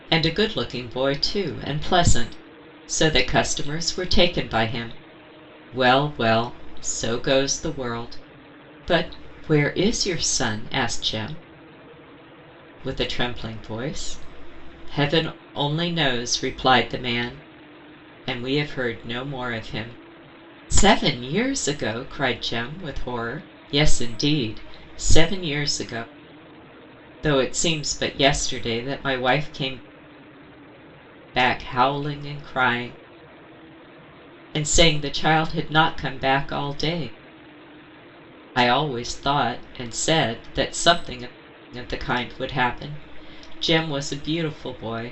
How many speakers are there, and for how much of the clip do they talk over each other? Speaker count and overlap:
1, no overlap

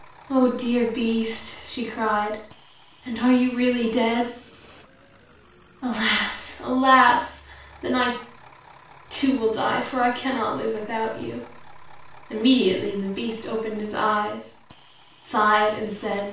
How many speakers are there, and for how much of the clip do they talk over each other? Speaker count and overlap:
1, no overlap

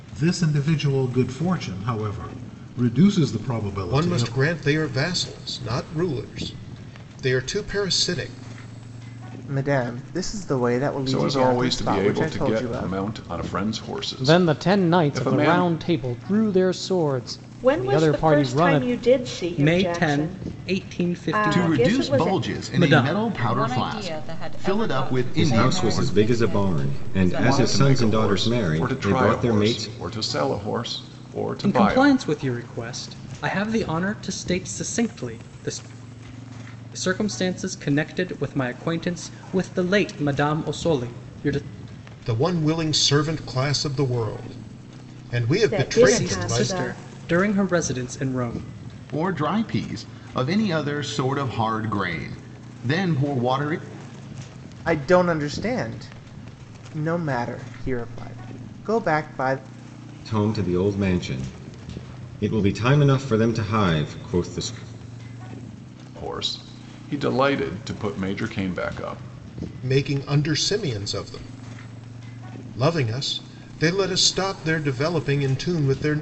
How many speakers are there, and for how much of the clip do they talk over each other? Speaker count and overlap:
10, about 23%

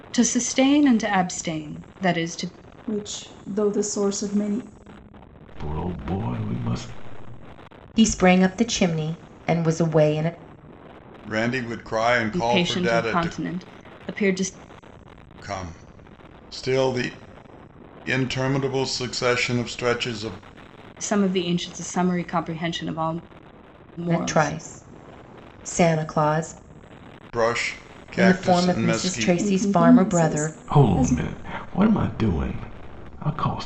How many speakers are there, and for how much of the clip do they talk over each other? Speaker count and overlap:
5, about 13%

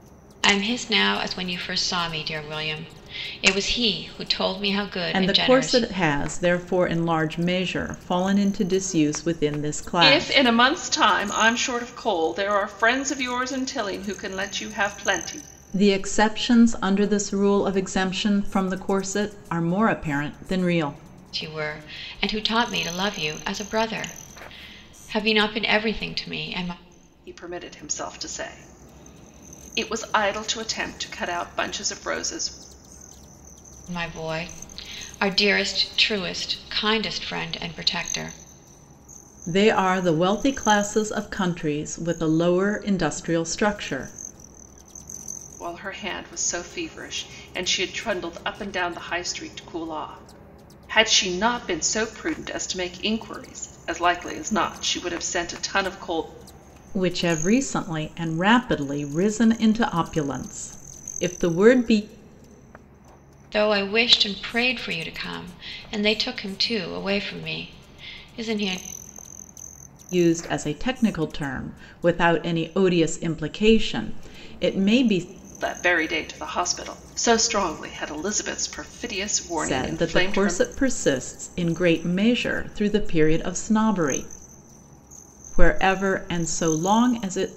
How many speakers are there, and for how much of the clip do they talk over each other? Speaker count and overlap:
3, about 3%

